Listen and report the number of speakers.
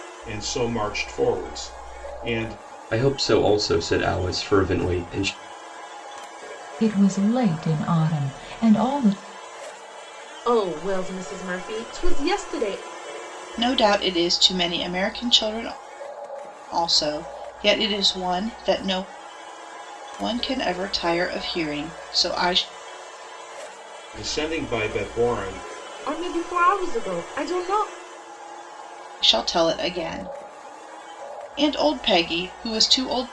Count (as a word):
five